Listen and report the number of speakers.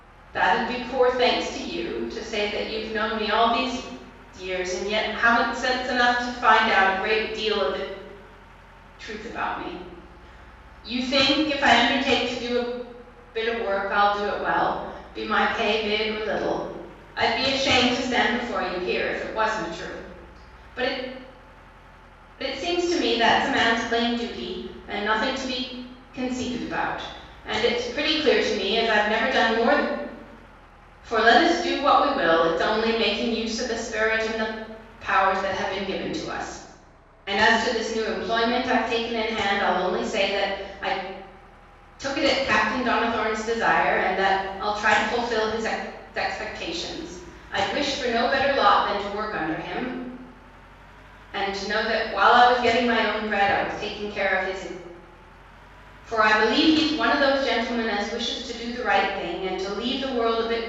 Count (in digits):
1